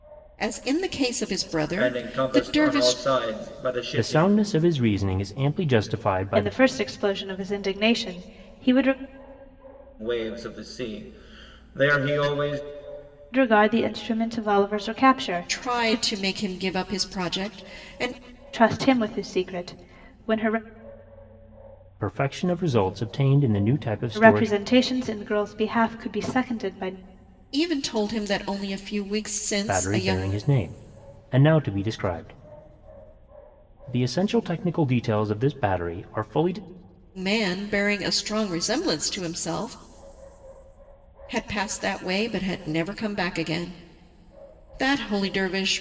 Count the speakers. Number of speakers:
four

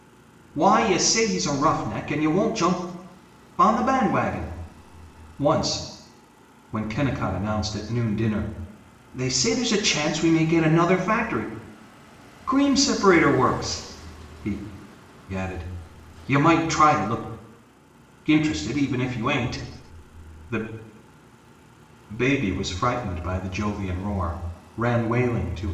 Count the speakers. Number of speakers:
one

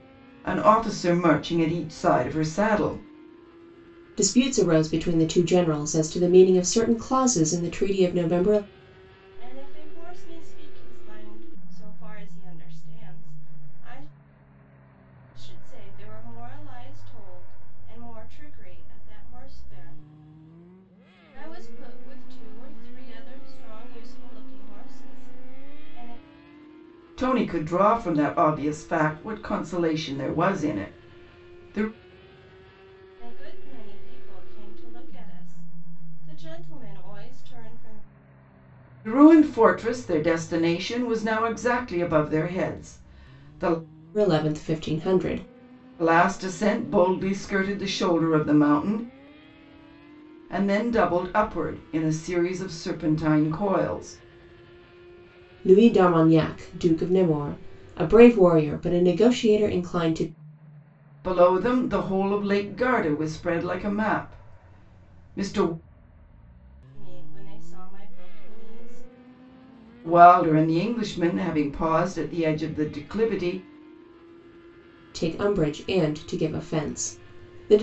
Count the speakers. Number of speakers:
three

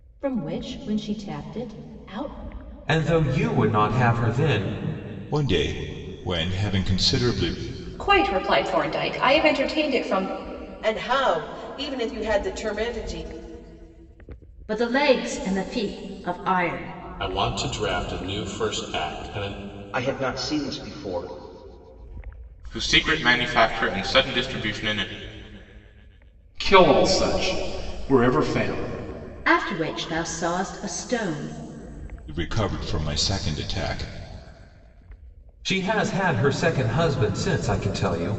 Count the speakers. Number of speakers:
ten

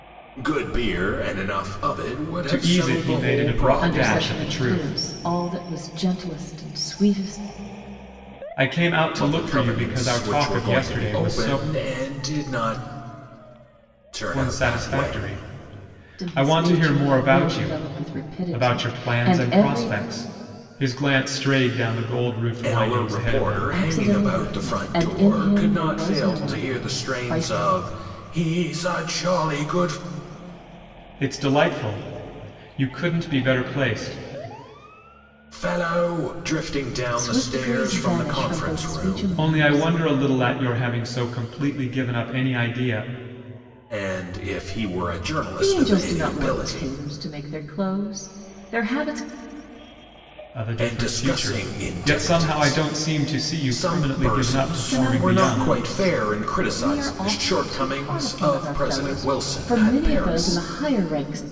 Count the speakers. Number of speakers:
three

